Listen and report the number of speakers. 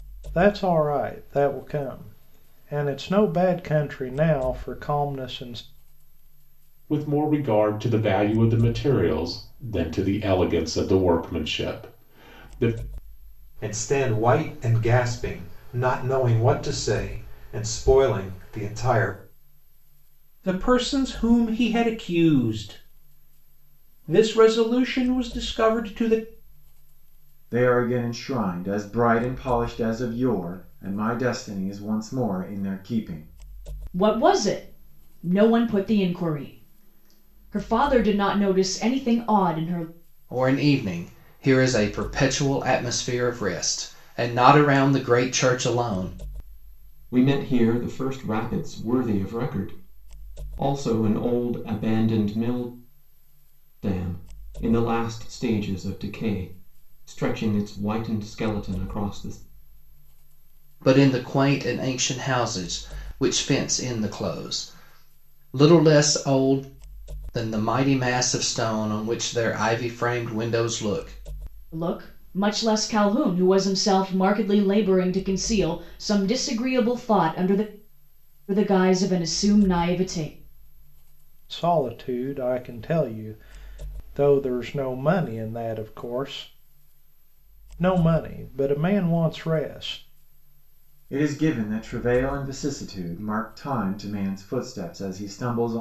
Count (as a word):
eight